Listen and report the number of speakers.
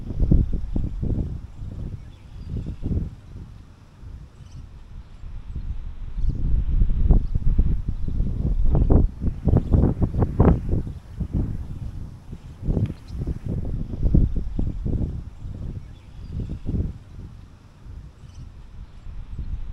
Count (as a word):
zero